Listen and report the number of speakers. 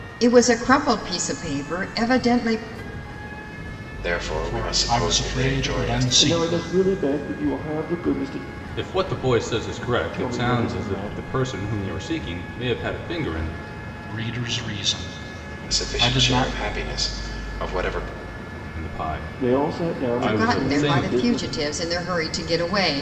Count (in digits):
5